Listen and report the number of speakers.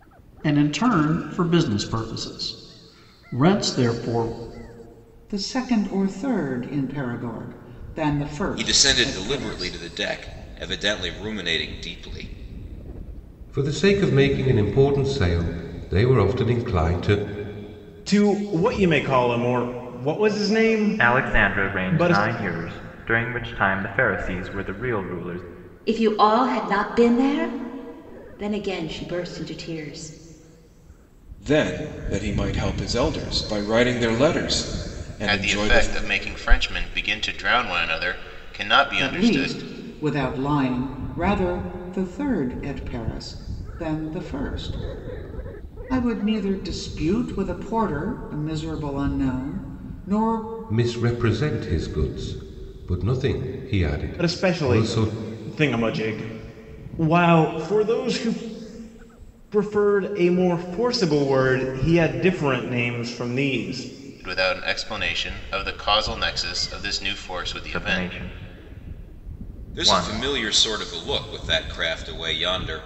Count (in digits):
9